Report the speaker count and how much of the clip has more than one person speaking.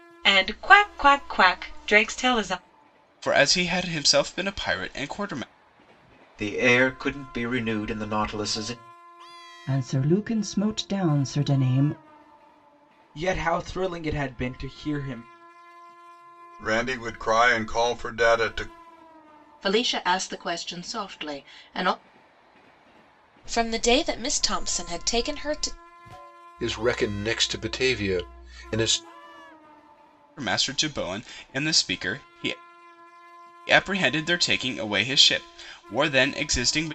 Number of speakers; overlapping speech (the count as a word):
nine, no overlap